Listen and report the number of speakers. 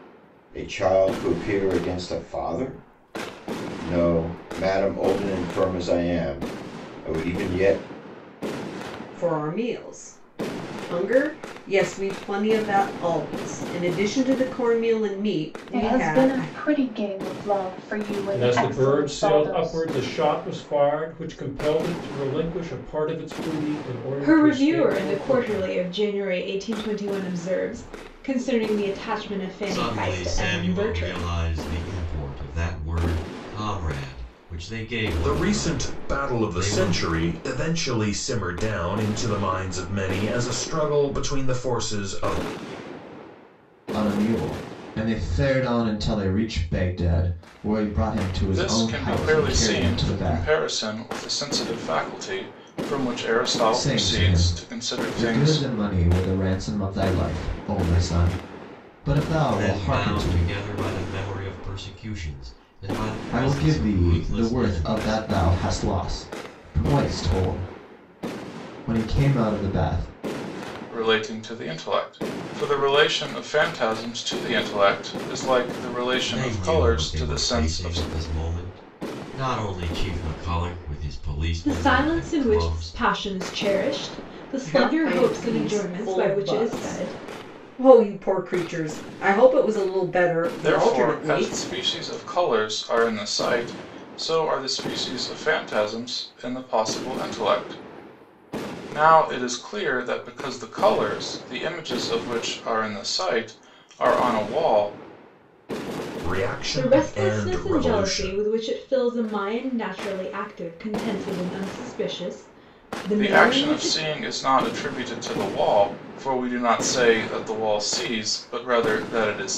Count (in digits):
9